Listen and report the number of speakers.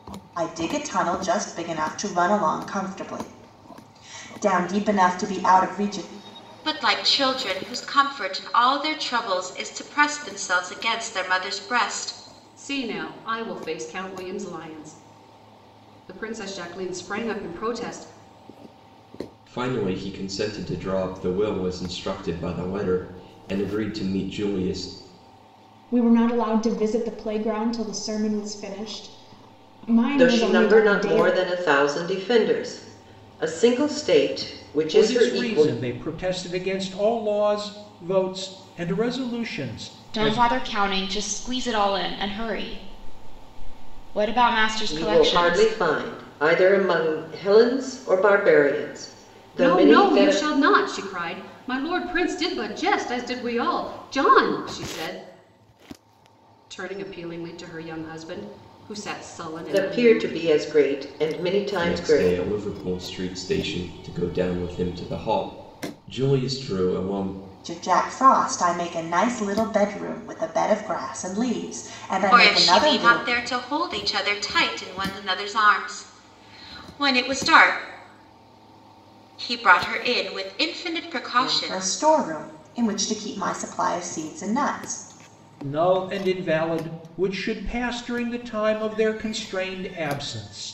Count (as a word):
eight